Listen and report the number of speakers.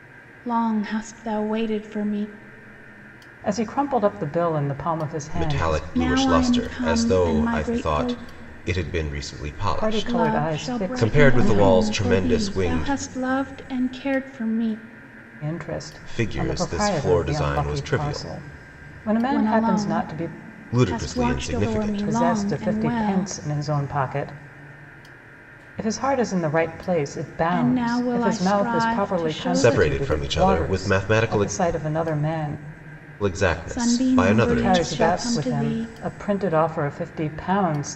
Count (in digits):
3